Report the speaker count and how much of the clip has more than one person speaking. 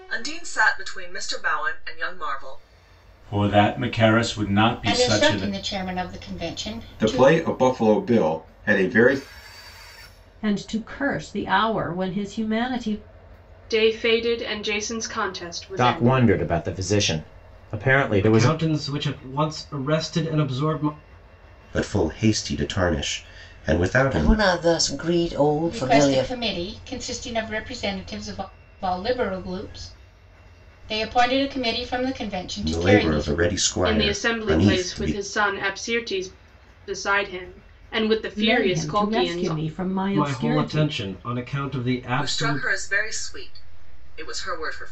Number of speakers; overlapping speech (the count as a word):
ten, about 17%